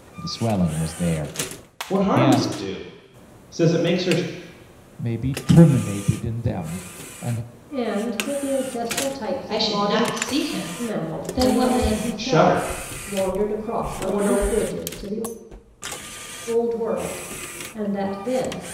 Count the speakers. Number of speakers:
5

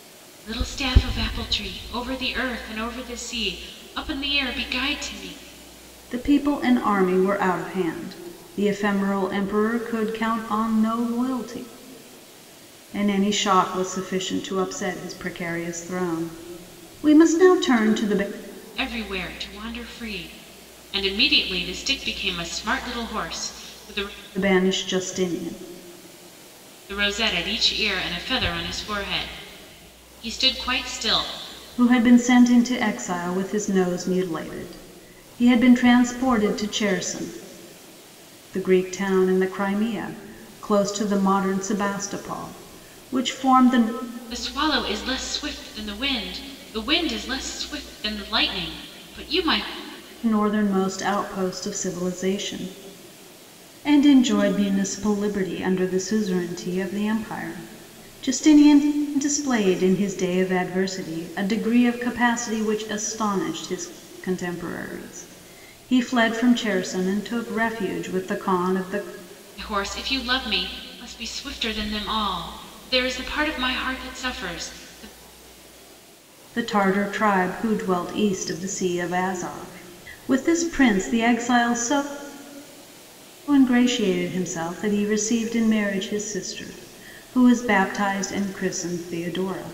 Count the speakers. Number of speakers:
2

